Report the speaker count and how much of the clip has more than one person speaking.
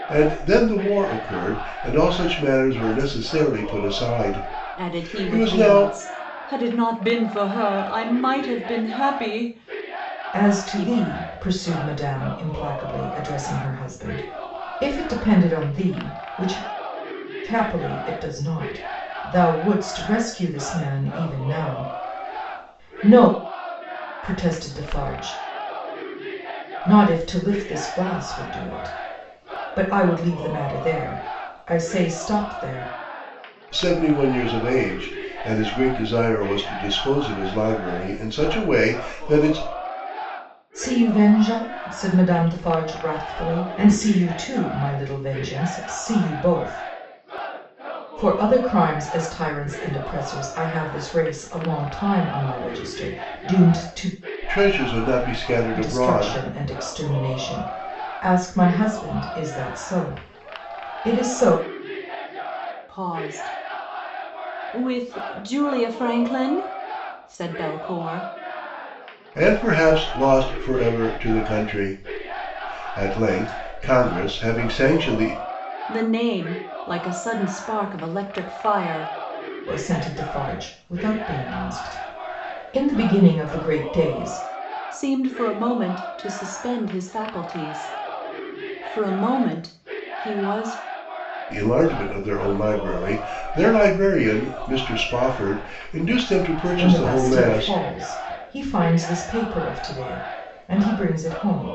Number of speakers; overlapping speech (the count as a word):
three, about 3%